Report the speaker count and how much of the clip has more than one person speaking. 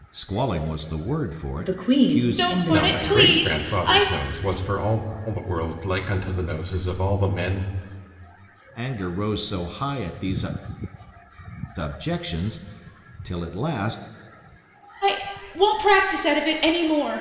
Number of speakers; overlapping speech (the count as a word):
four, about 15%